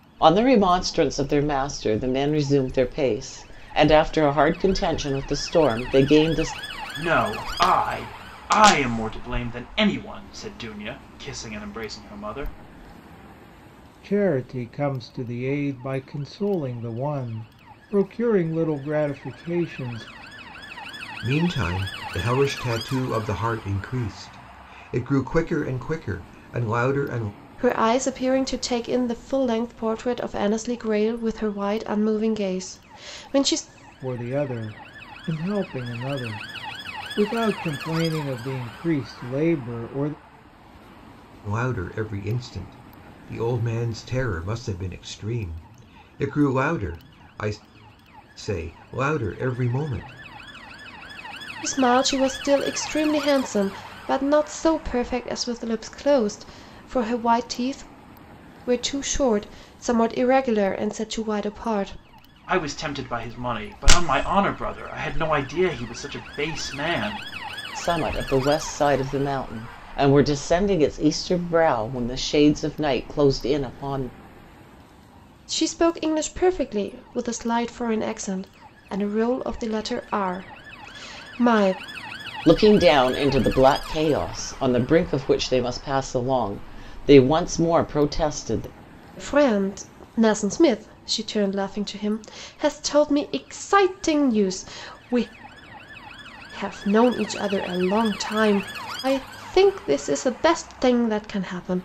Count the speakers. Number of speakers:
five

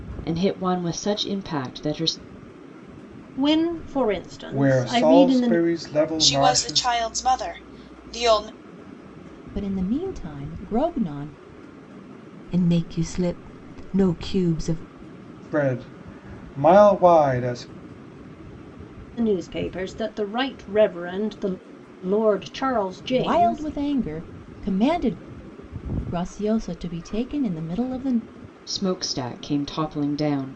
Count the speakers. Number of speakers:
six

